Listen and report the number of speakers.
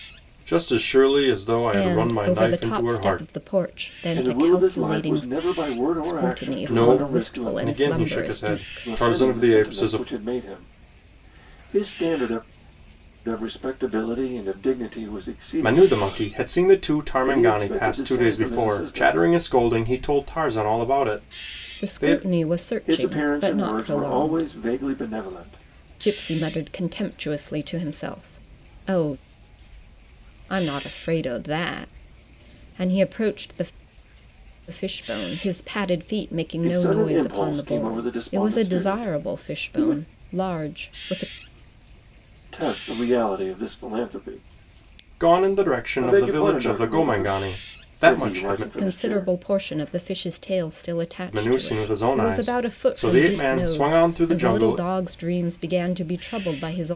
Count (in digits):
3